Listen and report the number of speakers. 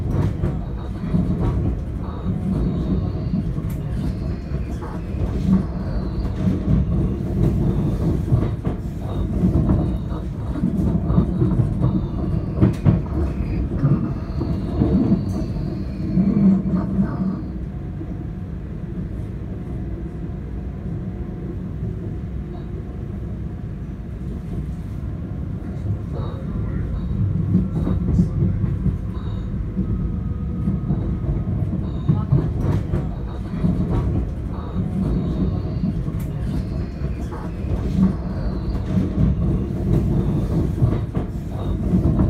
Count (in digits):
0